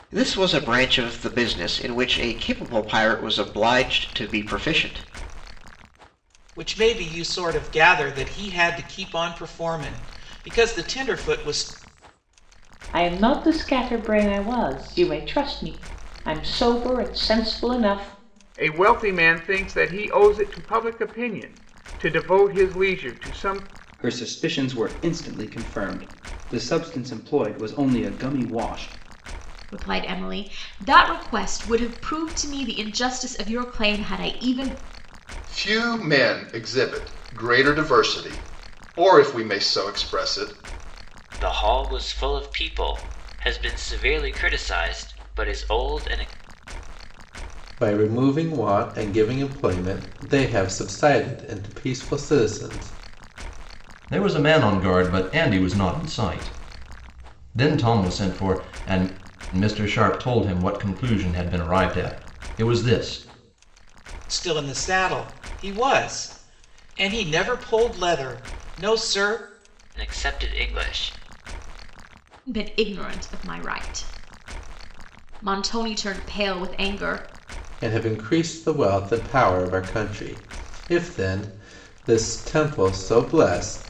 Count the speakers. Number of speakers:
10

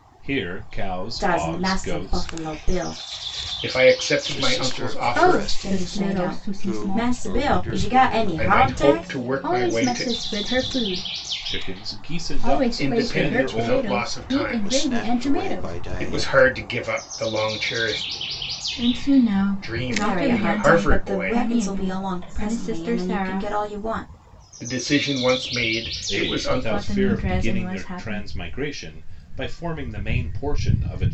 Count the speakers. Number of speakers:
5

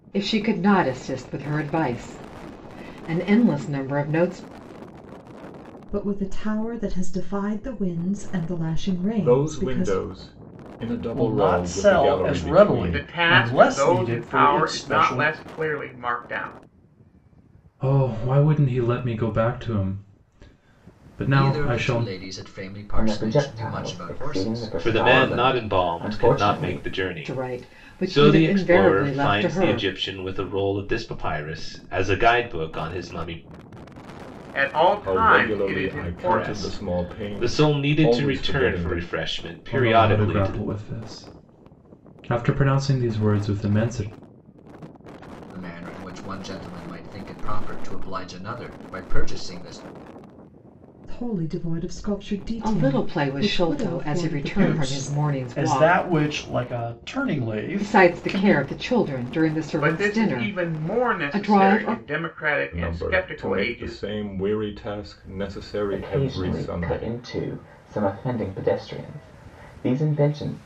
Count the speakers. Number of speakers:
9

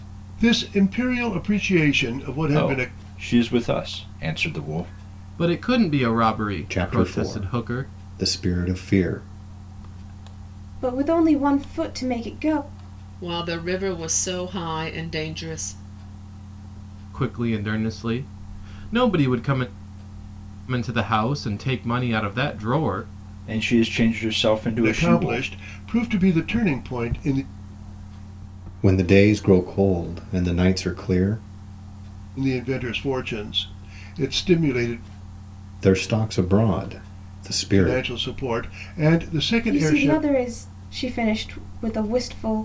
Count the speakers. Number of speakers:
6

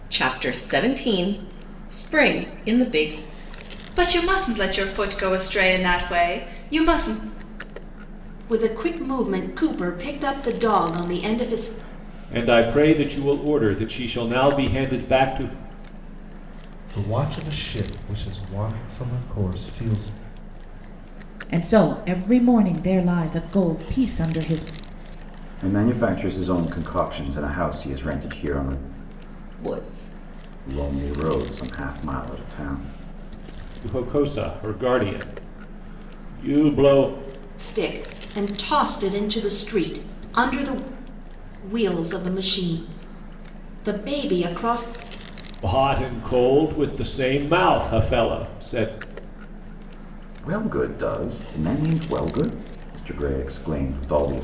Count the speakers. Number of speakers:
7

